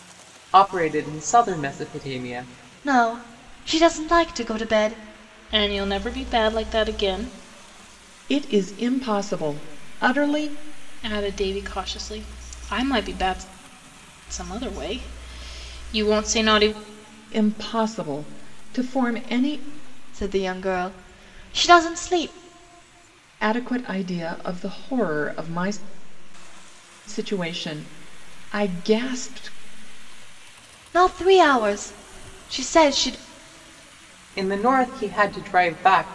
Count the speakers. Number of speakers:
4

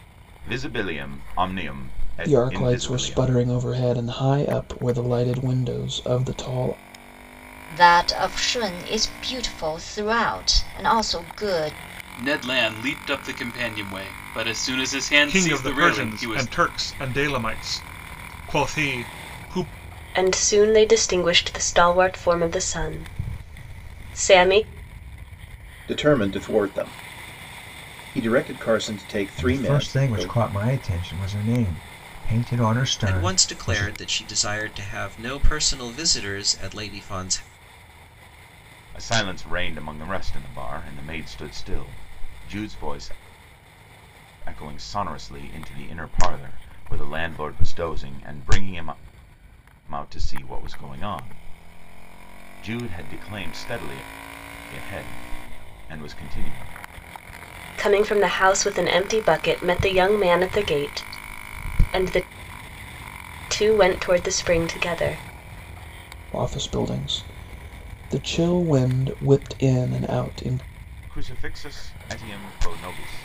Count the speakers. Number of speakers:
9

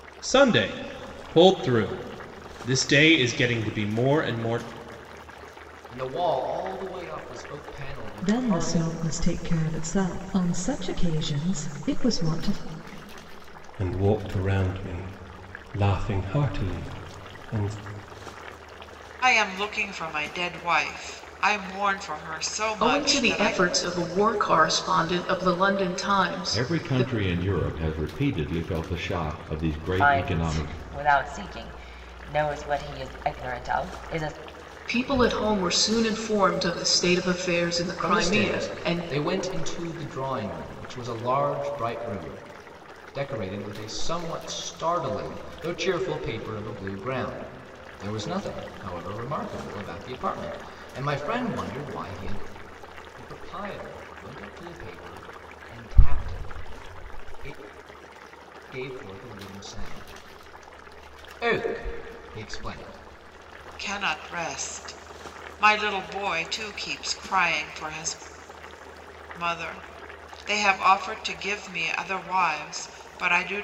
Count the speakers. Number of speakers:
8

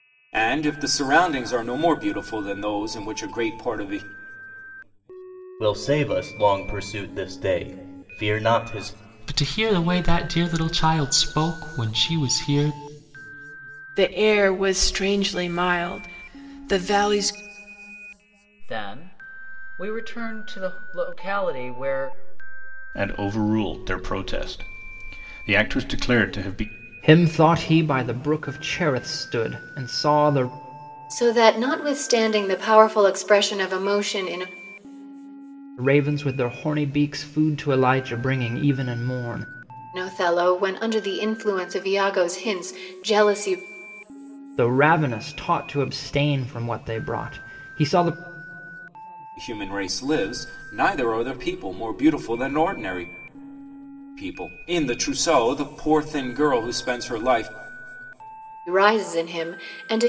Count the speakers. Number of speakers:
8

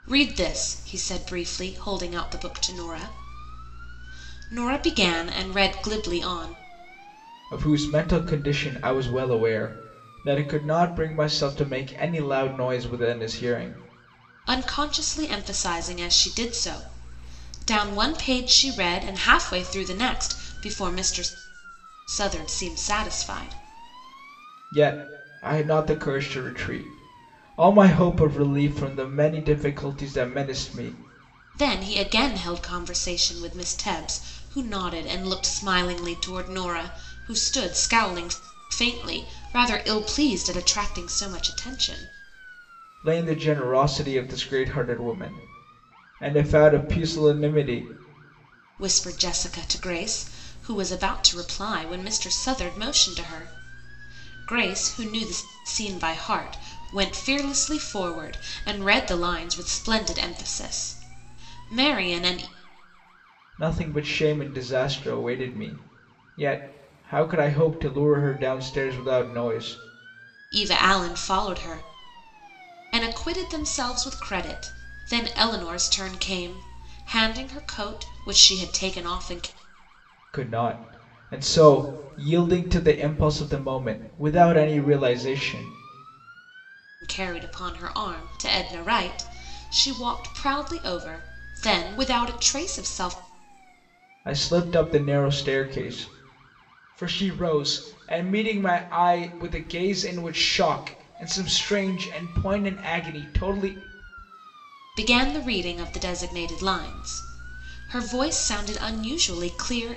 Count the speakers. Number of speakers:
2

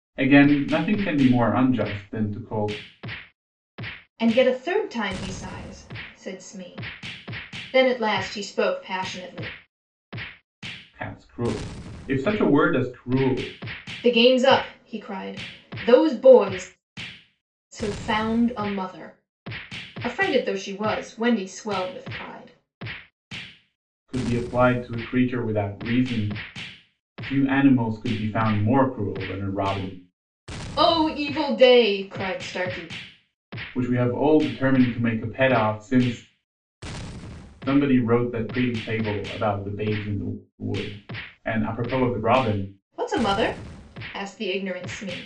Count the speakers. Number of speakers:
2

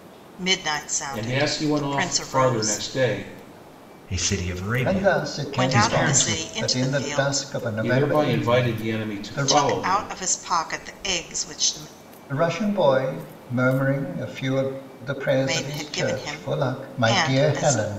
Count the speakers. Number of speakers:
4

